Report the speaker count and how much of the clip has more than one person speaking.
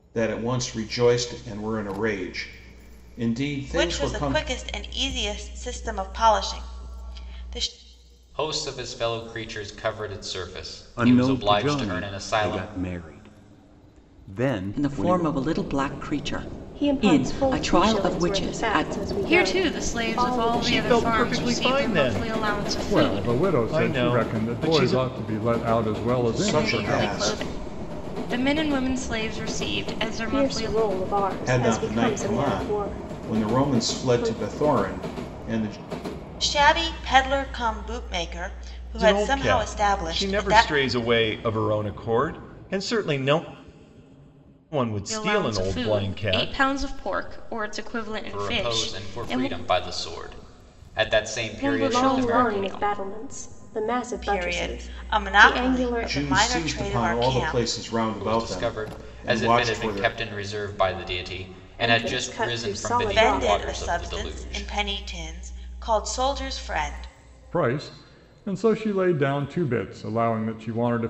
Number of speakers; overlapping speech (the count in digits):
9, about 42%